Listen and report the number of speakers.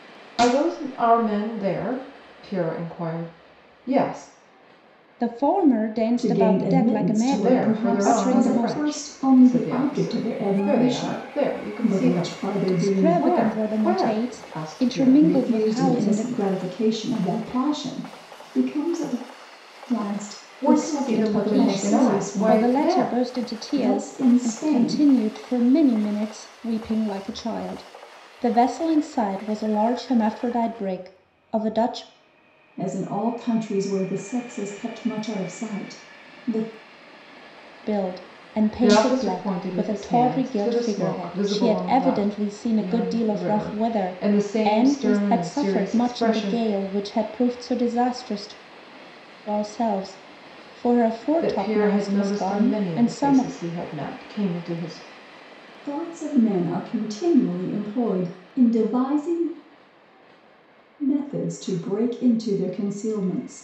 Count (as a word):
three